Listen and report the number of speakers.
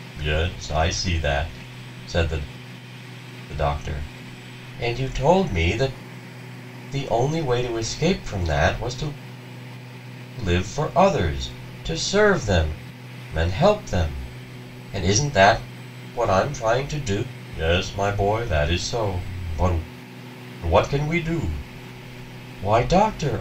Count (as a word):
one